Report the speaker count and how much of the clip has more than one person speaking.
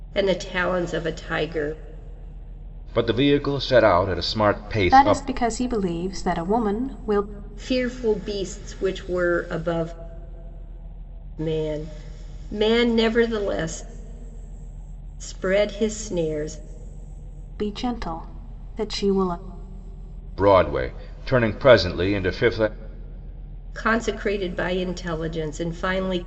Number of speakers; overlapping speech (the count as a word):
three, about 2%